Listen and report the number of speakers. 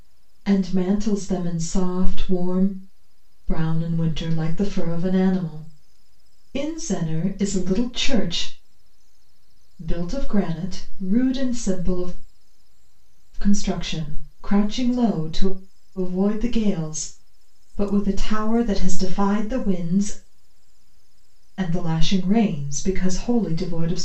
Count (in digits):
1